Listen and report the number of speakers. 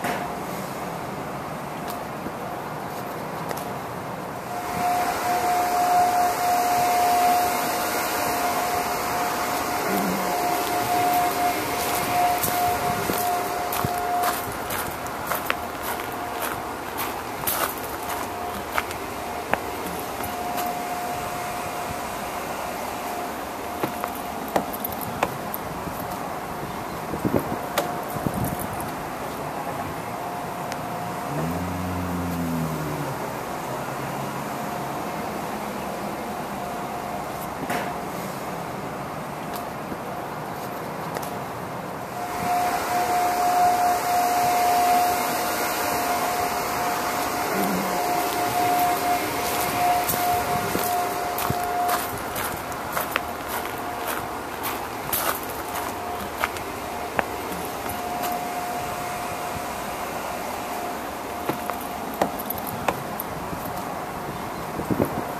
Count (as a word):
zero